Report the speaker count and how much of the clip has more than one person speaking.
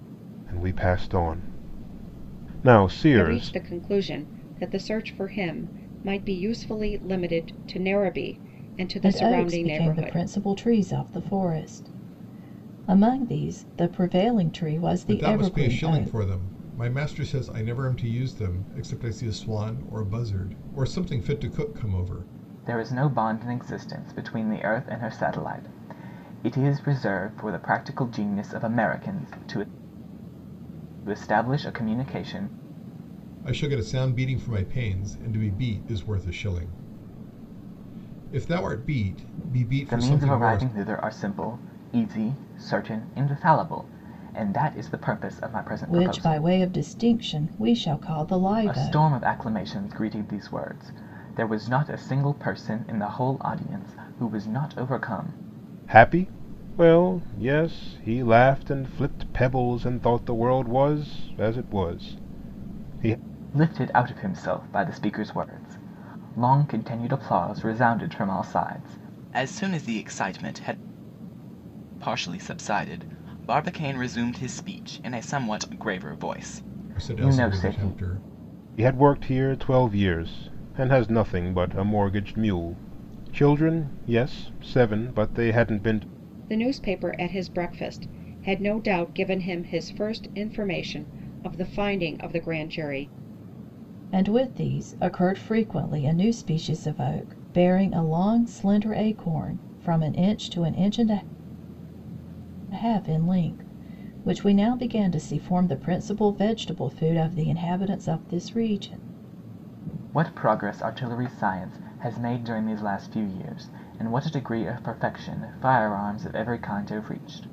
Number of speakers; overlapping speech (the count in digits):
5, about 5%